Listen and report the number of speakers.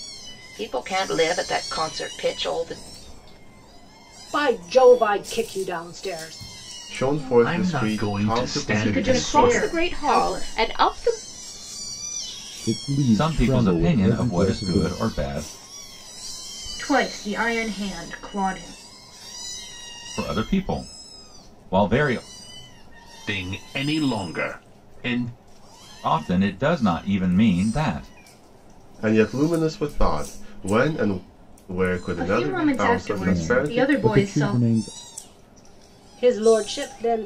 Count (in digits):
8